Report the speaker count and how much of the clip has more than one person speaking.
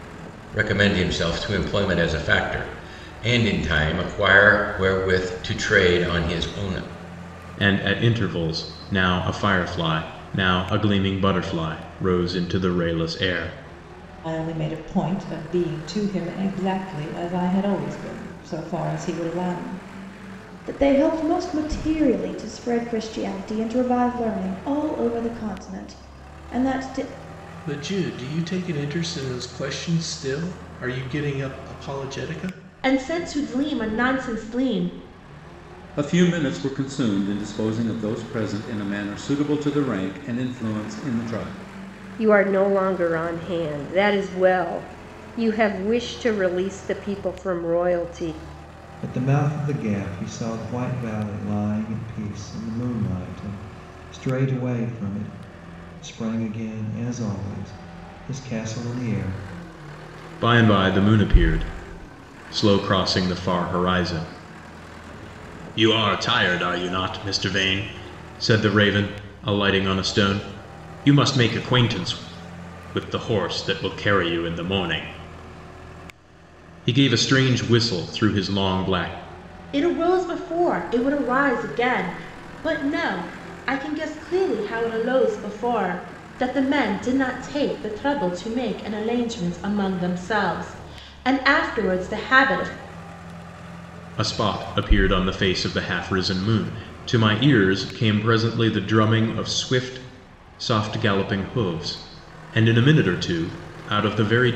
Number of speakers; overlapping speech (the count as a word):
nine, no overlap